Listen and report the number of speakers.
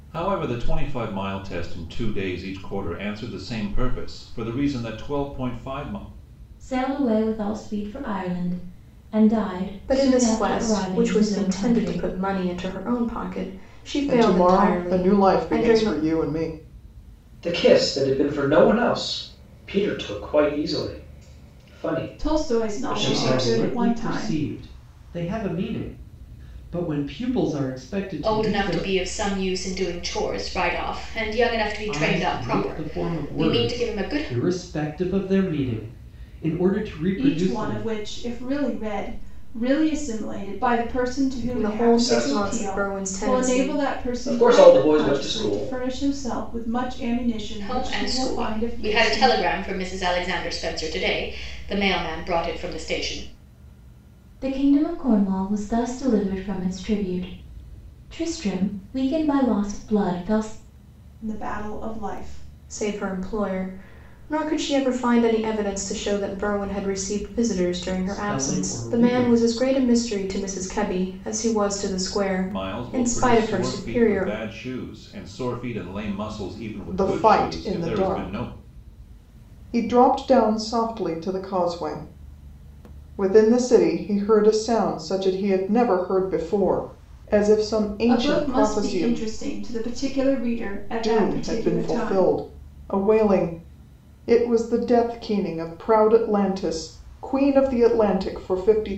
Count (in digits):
8